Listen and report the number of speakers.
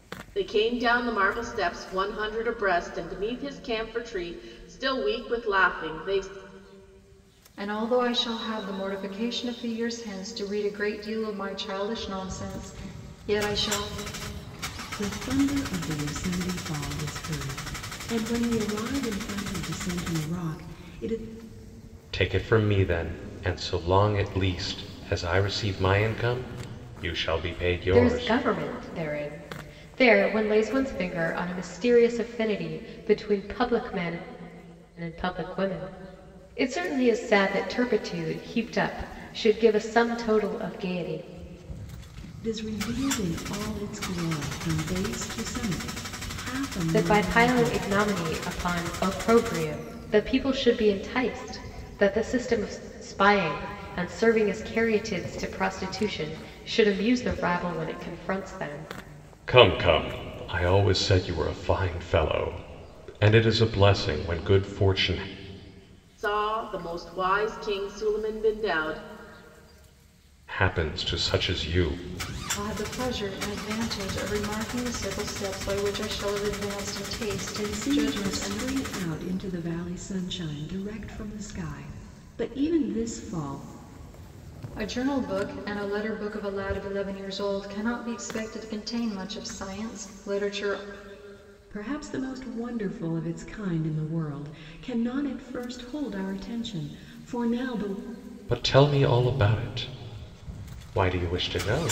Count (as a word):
five